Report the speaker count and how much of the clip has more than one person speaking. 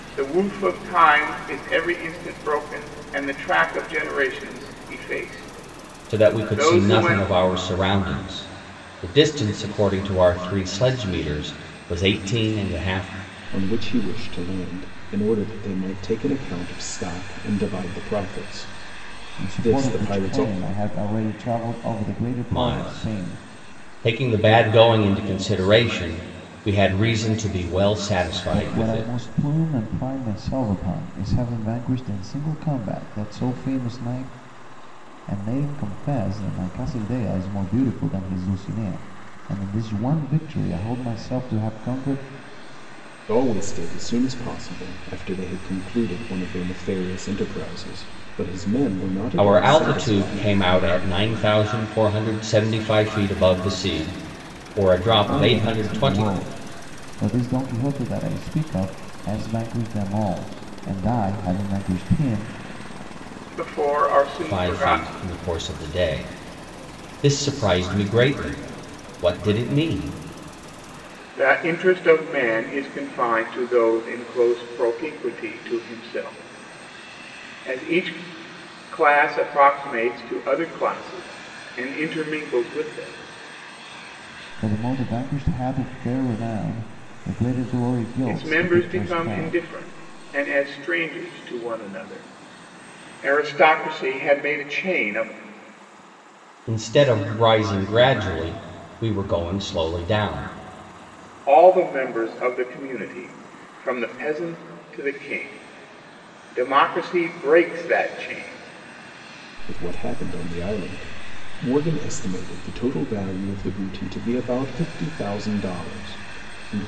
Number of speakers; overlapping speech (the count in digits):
4, about 7%